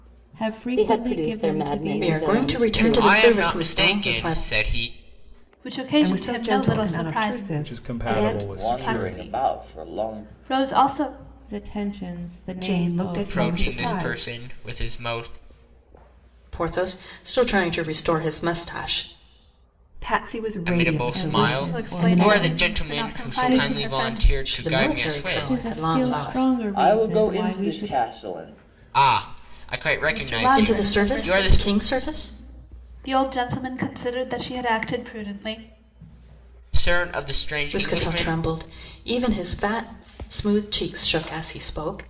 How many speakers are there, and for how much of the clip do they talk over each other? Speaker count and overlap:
eight, about 47%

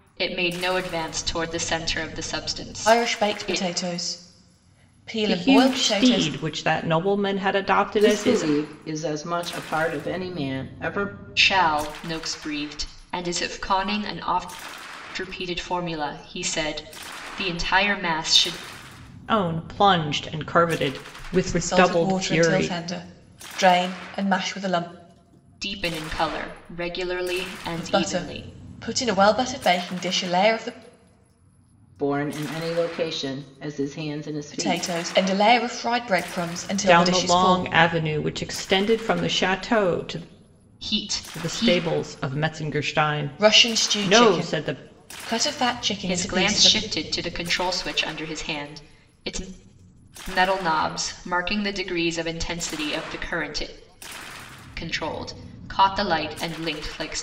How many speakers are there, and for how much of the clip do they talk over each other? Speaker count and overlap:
four, about 16%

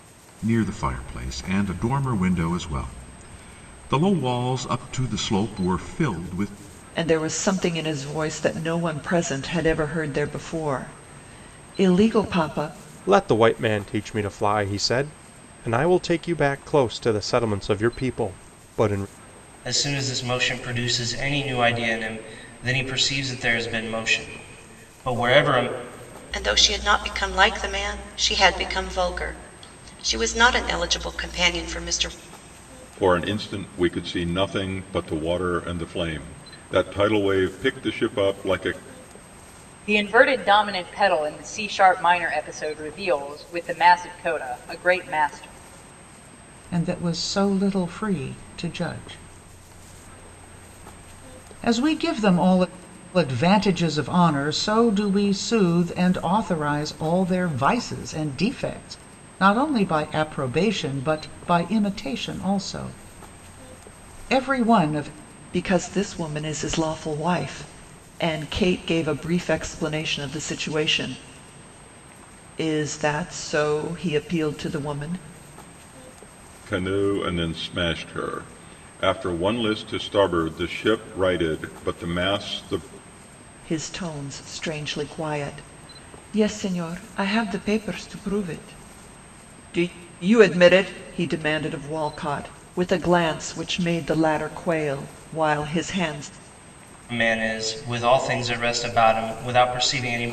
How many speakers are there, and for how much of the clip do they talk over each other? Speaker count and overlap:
eight, no overlap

